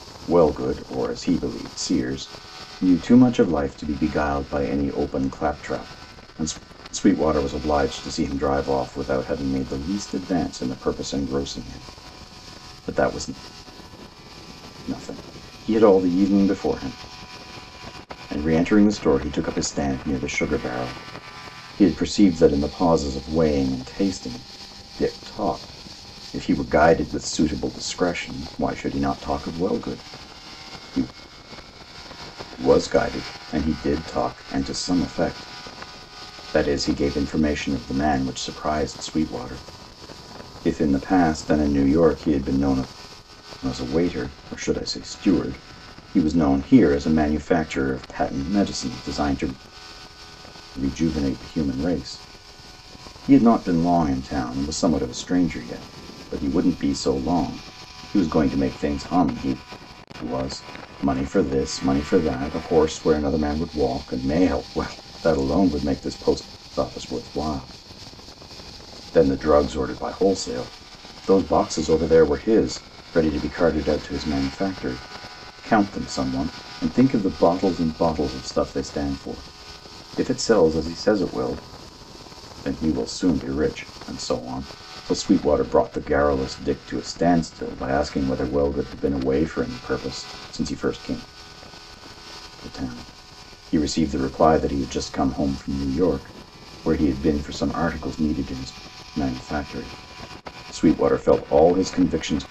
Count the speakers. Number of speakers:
one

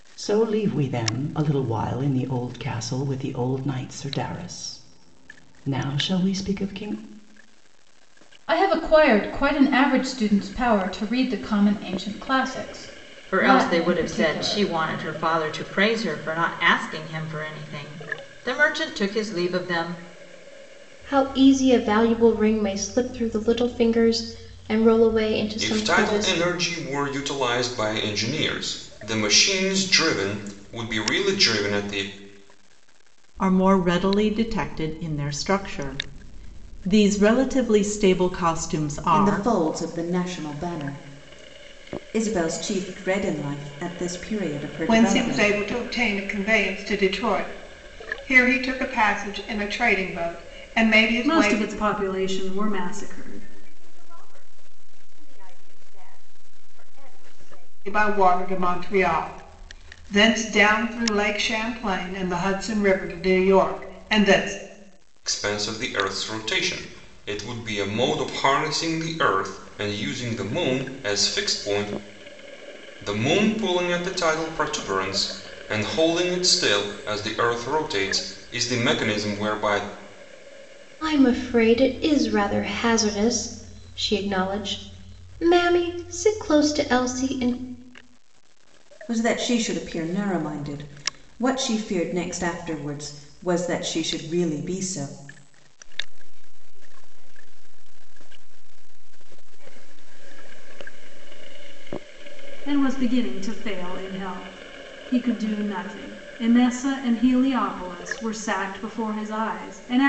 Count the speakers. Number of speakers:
ten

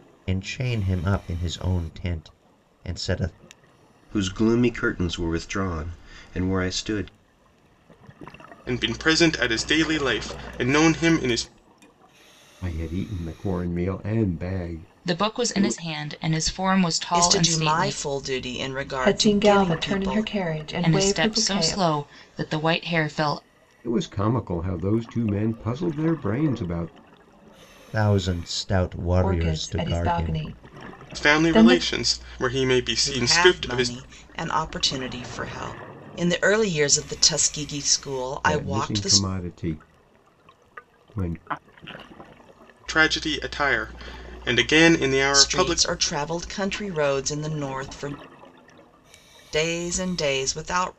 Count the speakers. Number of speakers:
seven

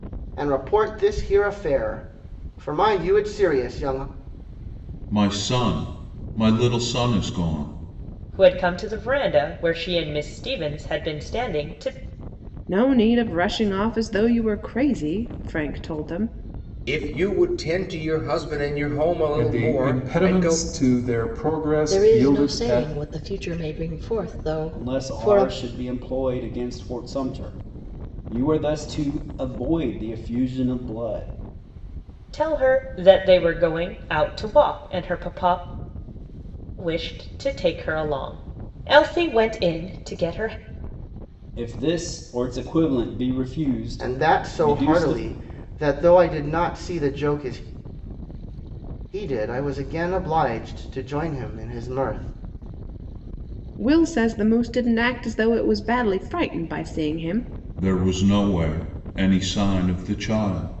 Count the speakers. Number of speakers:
eight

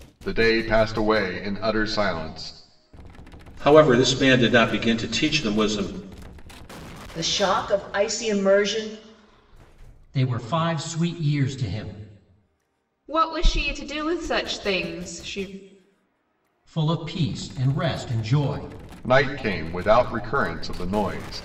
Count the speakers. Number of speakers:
five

